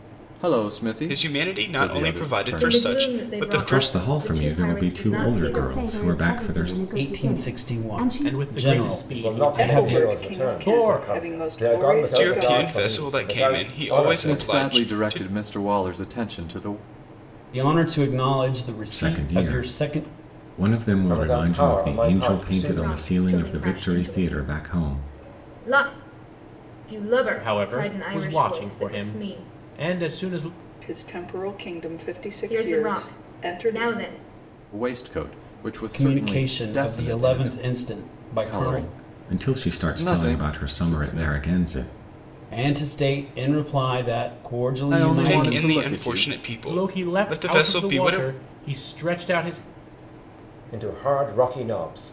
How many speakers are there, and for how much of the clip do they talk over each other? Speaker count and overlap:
nine, about 58%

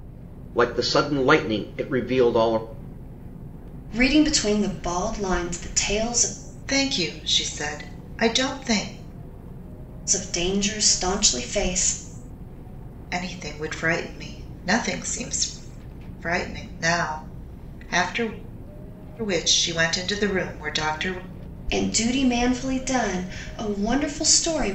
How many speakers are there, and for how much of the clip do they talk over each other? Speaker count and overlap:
three, no overlap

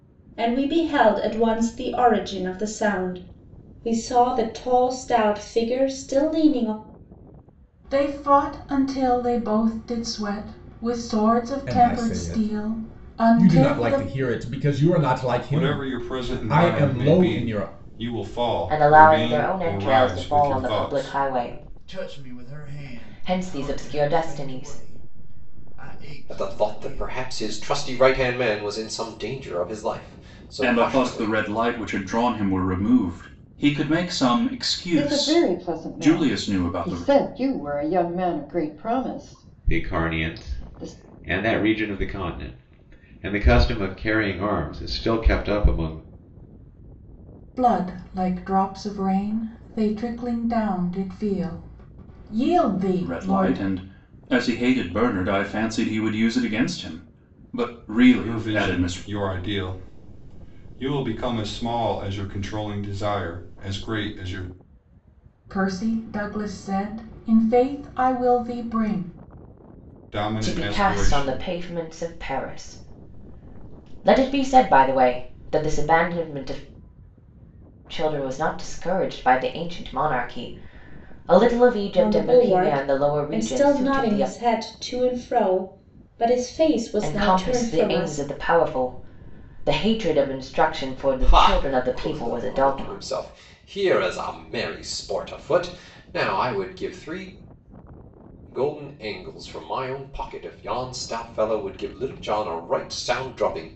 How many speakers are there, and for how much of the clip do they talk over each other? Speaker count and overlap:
ten, about 24%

